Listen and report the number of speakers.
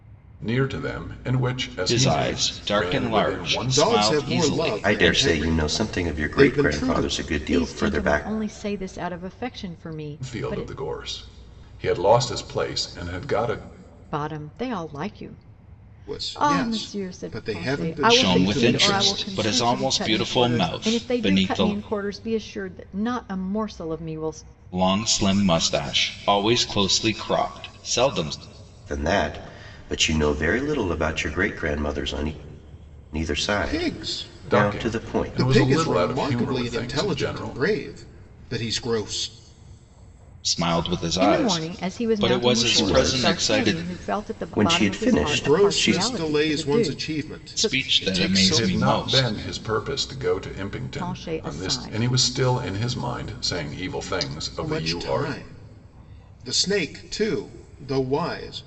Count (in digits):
5